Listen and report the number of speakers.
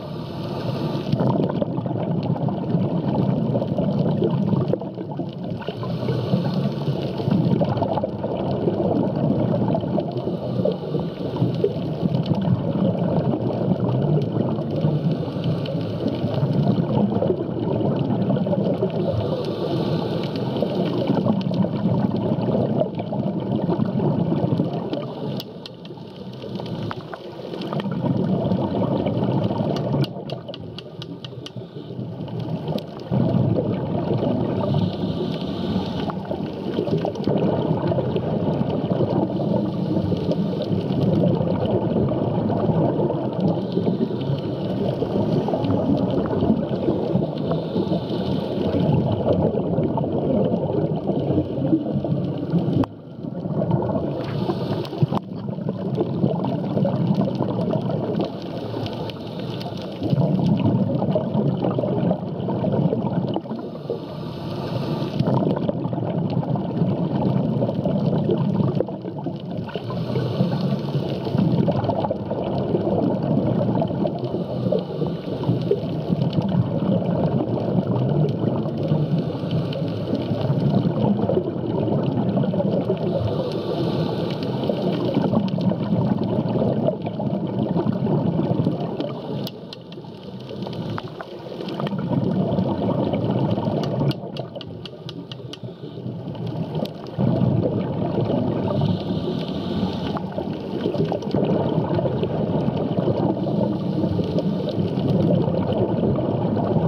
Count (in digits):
0